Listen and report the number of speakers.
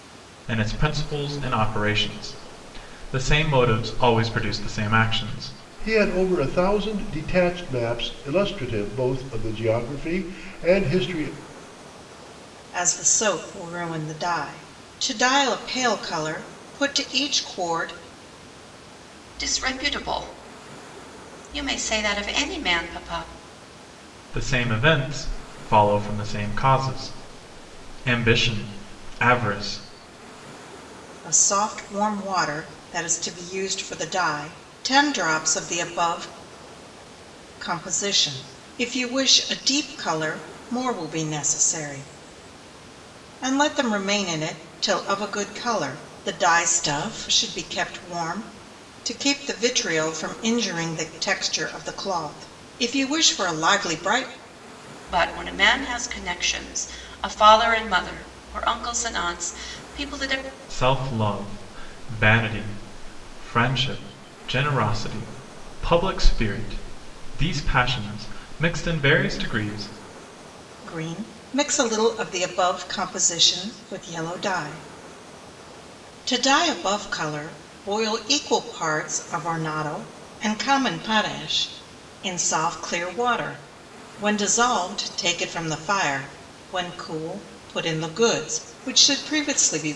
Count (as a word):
four